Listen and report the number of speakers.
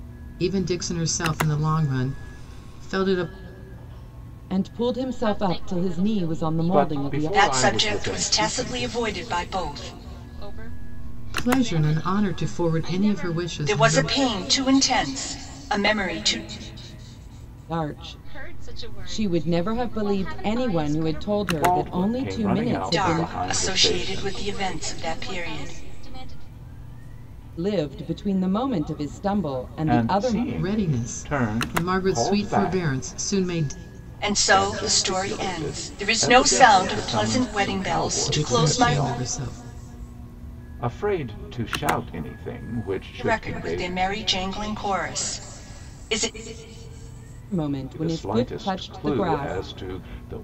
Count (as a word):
five